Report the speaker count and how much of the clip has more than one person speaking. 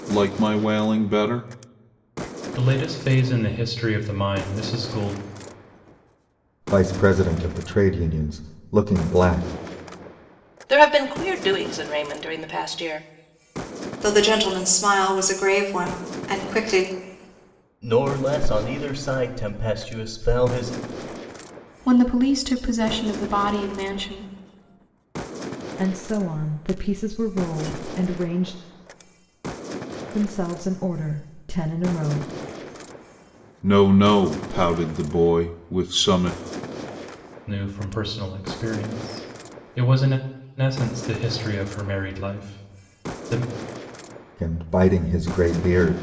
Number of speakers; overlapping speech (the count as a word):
eight, no overlap